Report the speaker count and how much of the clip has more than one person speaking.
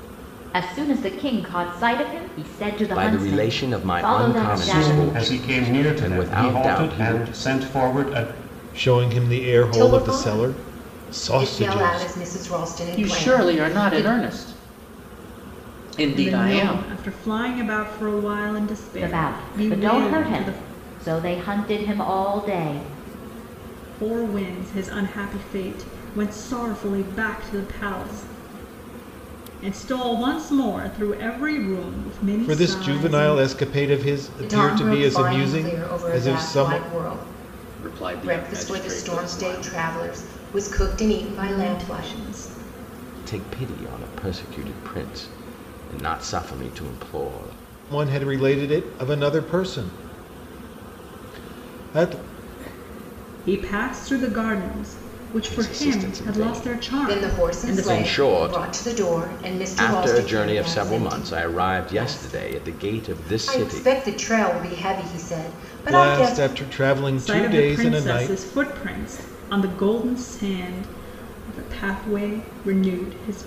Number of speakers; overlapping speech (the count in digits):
7, about 34%